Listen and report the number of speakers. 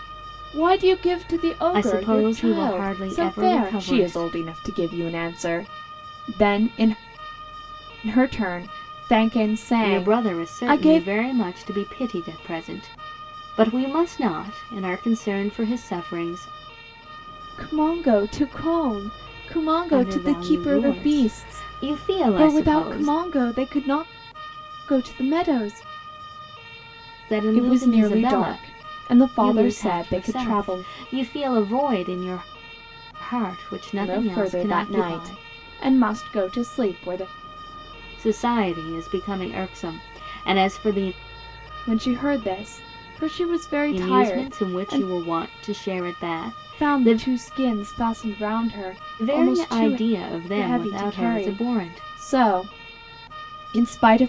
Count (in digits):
2